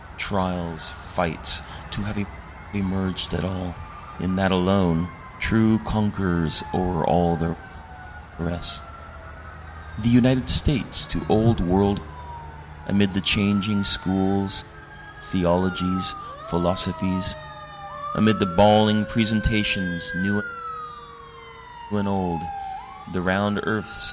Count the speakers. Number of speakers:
one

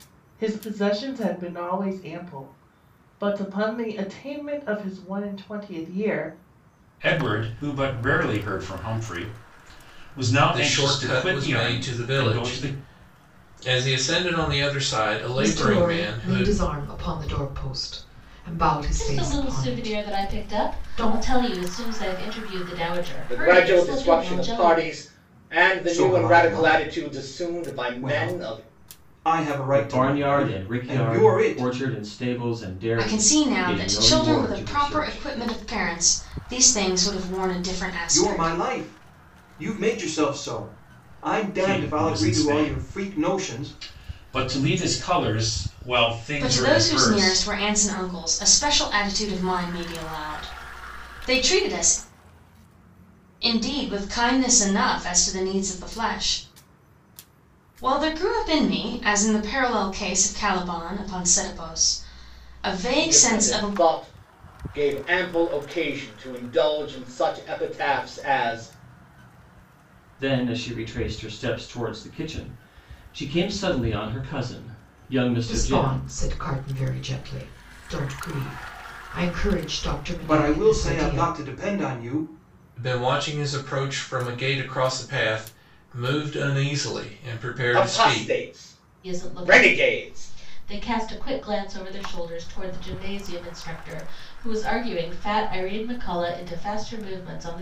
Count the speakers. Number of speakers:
nine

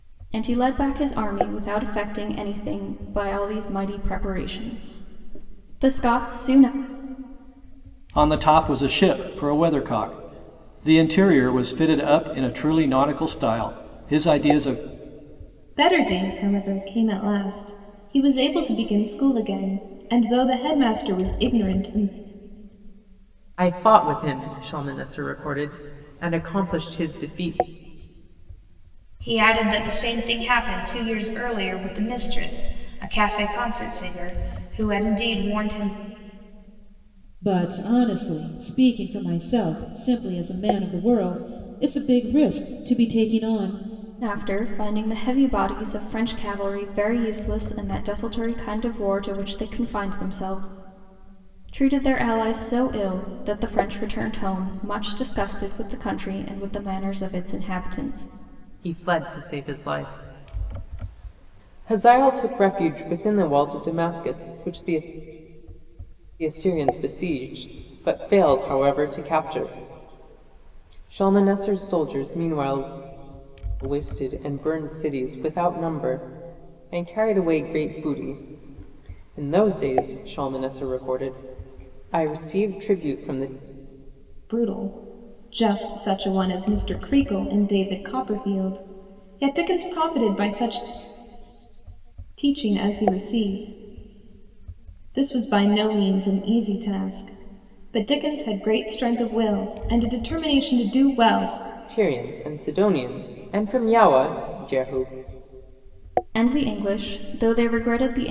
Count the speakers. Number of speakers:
six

